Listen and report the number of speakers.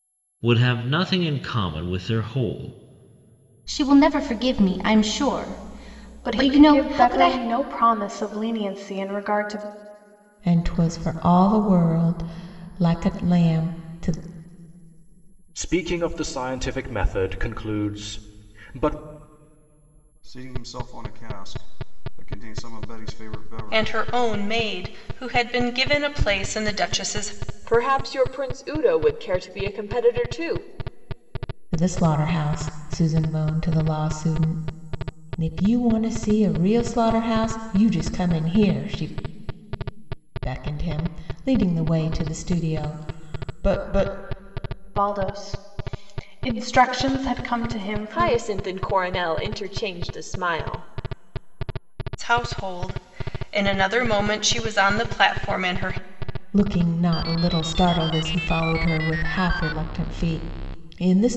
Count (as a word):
eight